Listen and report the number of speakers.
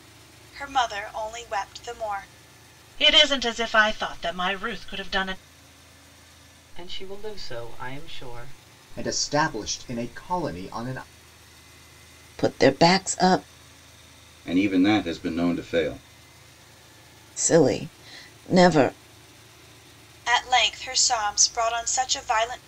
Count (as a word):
six